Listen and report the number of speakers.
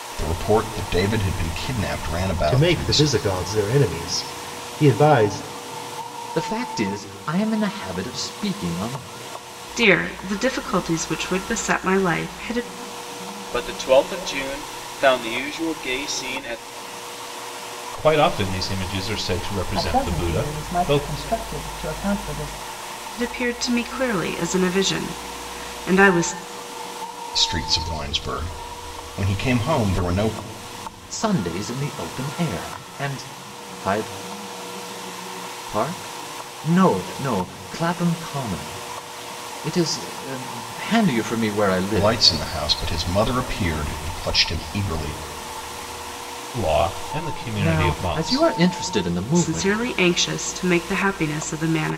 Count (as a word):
seven